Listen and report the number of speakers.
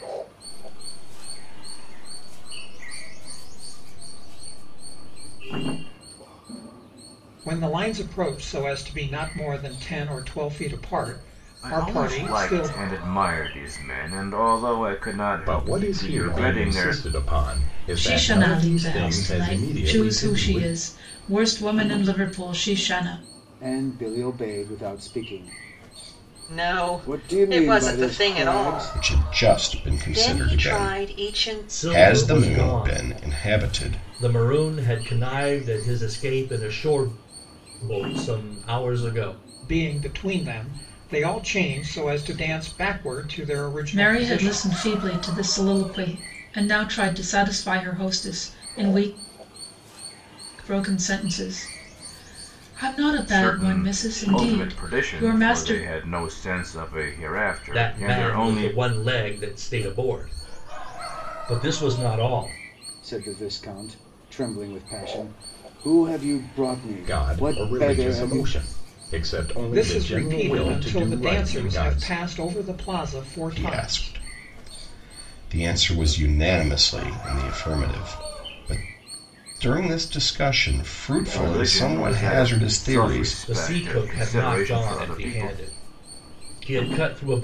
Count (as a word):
nine